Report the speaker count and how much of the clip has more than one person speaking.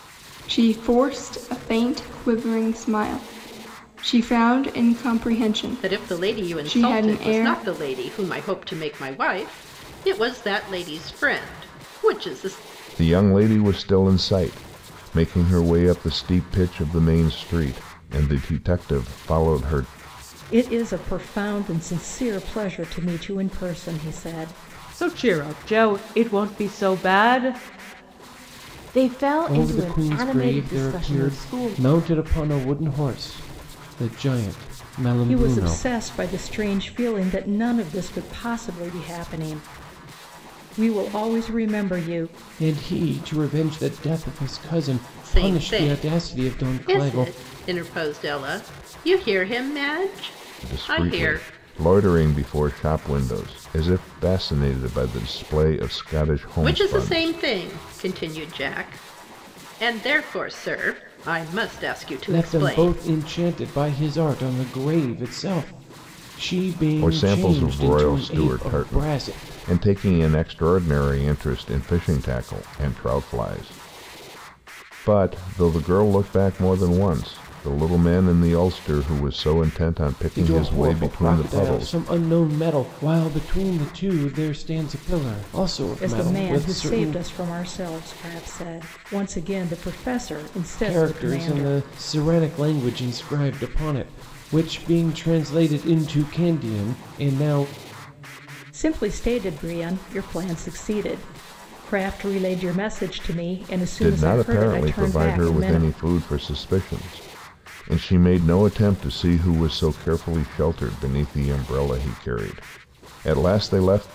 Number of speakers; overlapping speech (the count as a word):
six, about 15%